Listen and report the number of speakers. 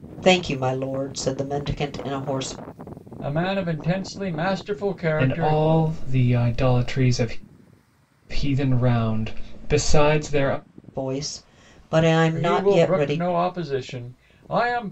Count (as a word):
three